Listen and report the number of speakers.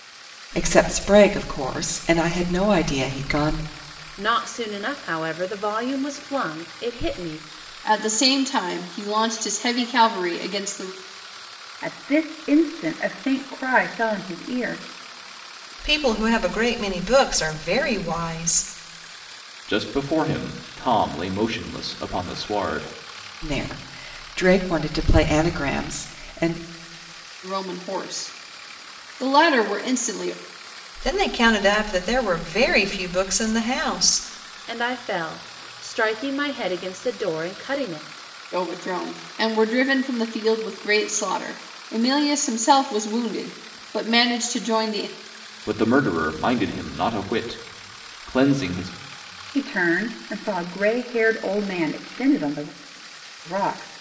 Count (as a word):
six